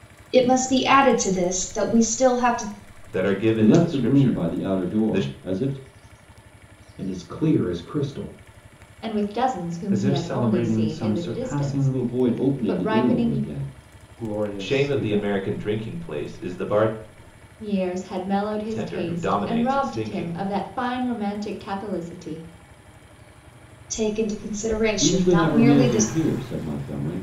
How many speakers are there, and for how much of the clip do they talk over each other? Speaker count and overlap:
6, about 34%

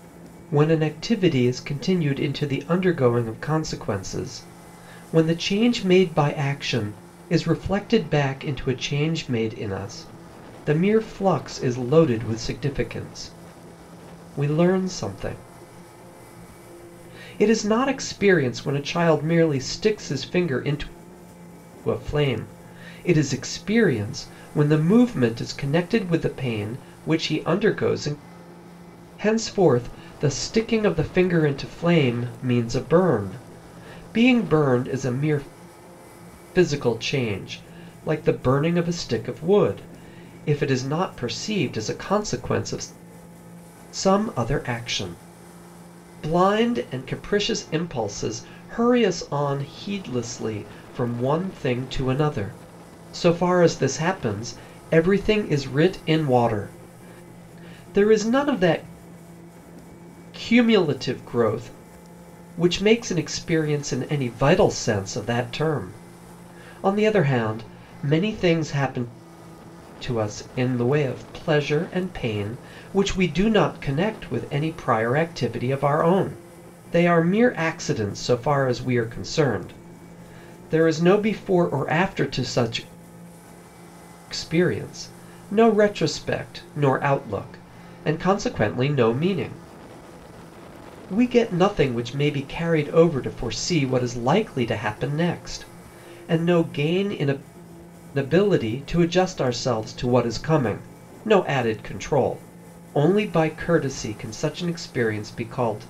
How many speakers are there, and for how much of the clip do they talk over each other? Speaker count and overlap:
1, no overlap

